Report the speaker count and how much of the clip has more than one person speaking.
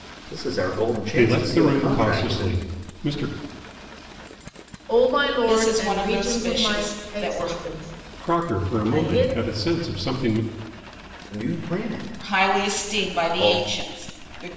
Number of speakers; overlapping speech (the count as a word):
four, about 41%